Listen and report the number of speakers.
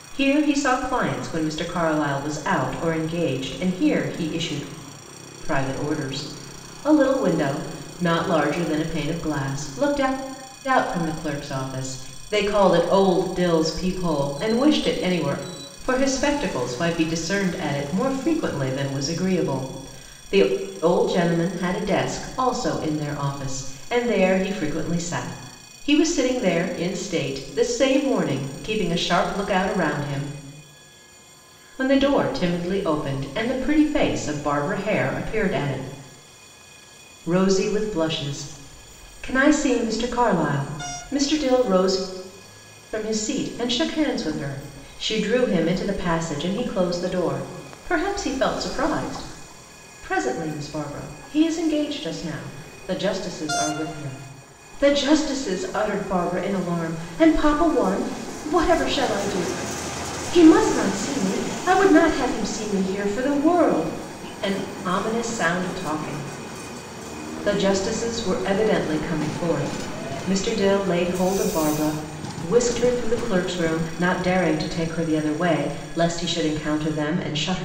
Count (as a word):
one